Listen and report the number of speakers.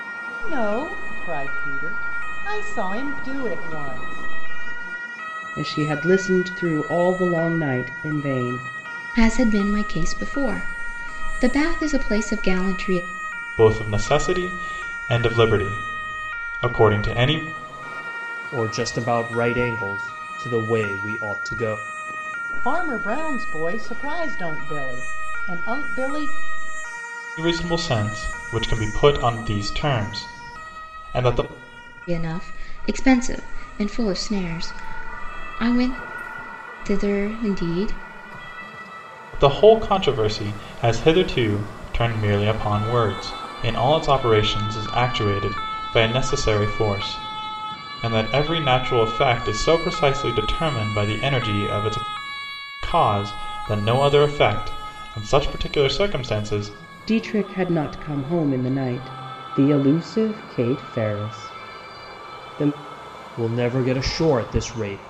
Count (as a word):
five